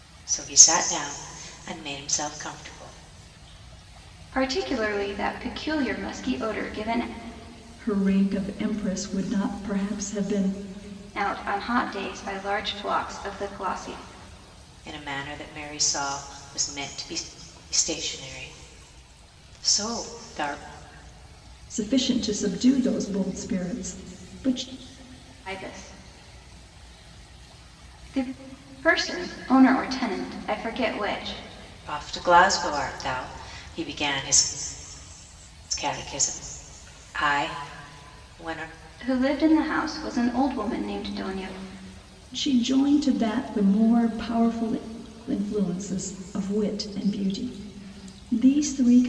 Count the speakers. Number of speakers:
three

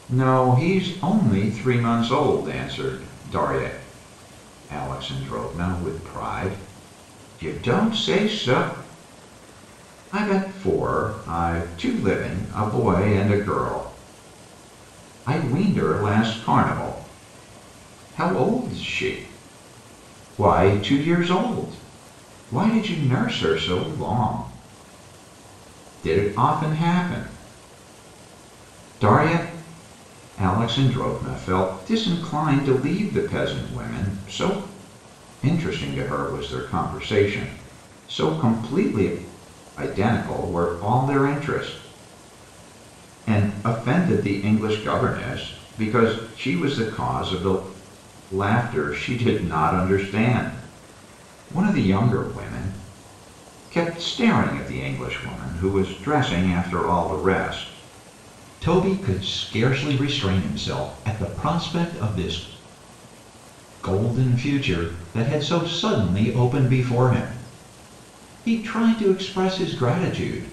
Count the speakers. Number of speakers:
one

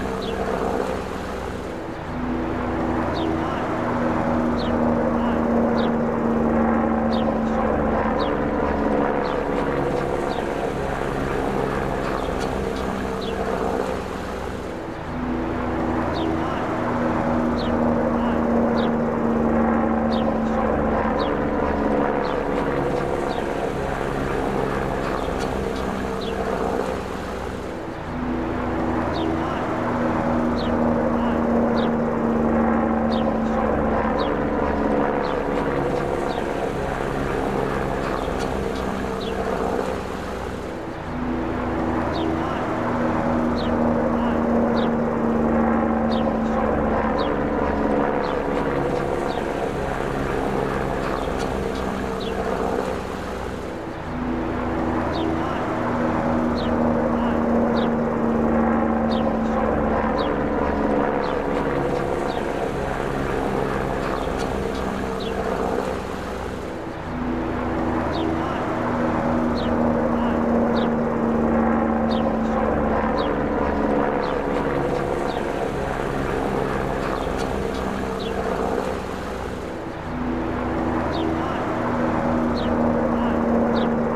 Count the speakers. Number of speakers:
zero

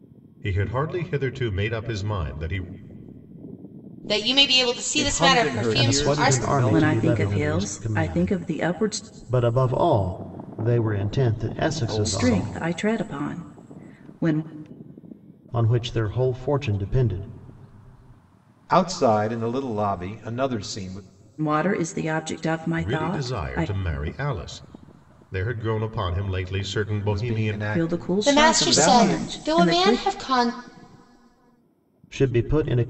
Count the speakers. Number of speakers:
five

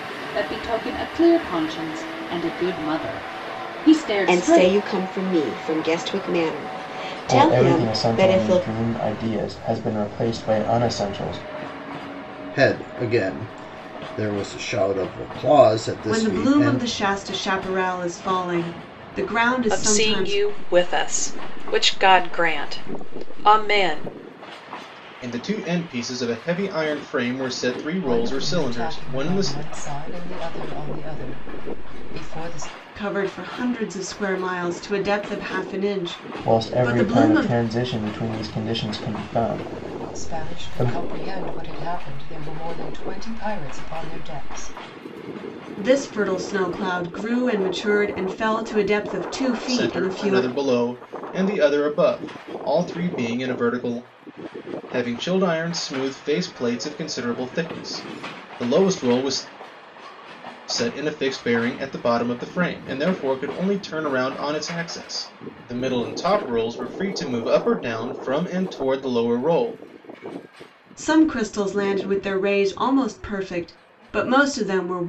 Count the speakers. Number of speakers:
eight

